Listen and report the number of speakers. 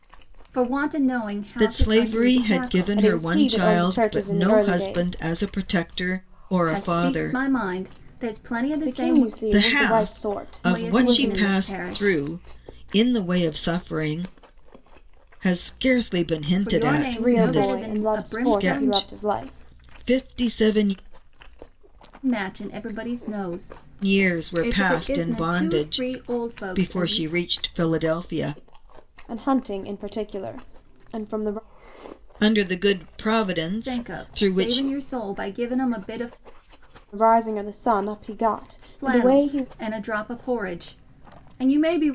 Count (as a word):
three